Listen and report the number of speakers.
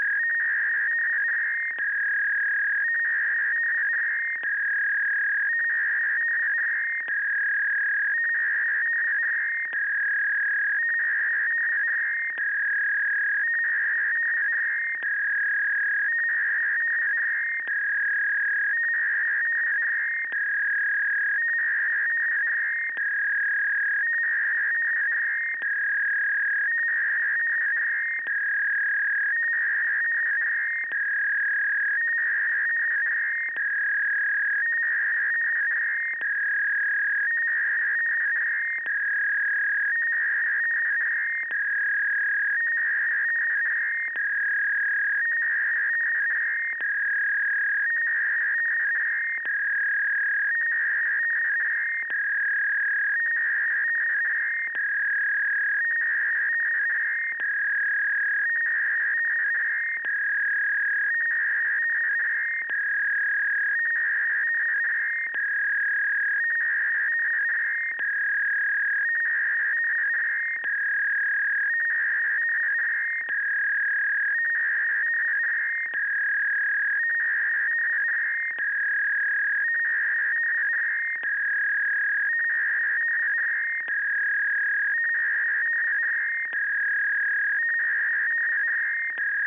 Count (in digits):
0